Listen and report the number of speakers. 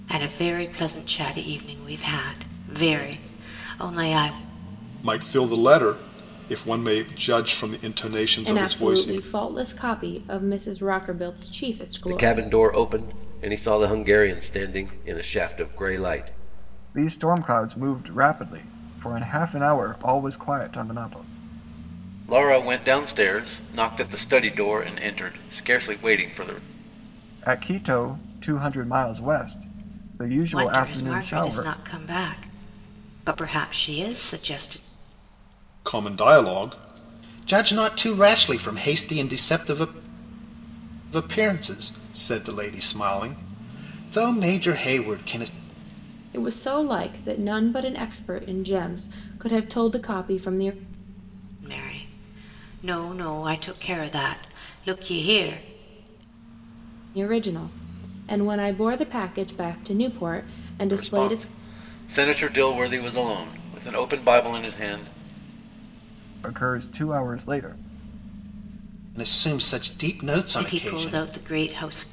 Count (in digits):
5